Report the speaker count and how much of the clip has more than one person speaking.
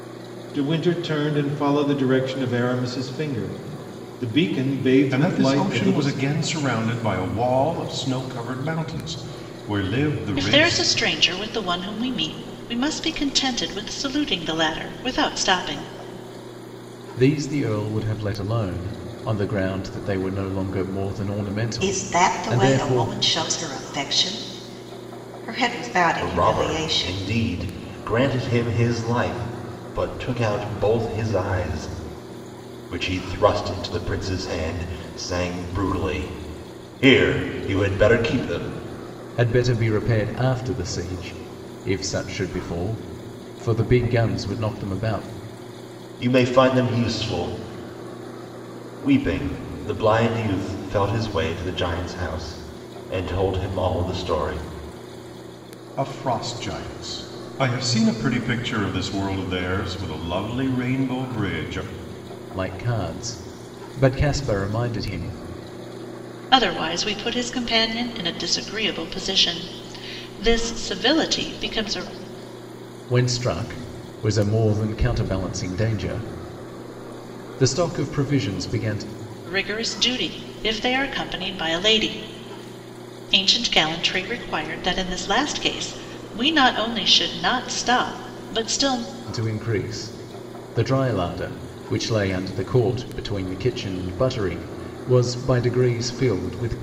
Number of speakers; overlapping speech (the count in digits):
6, about 4%